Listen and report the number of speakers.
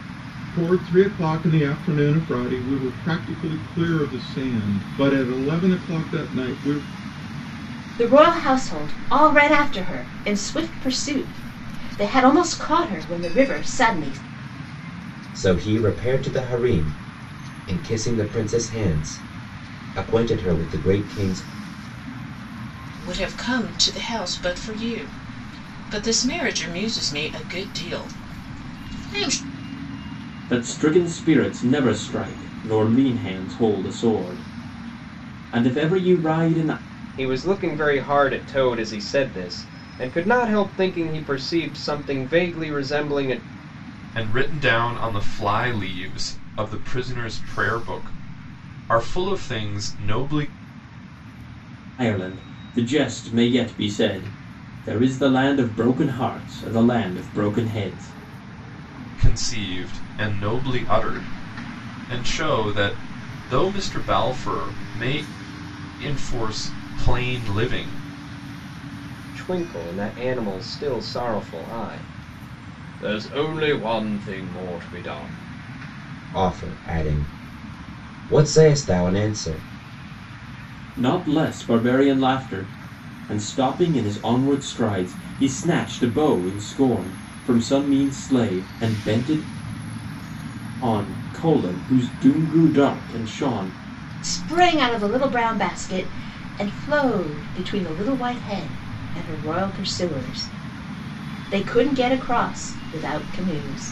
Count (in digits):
7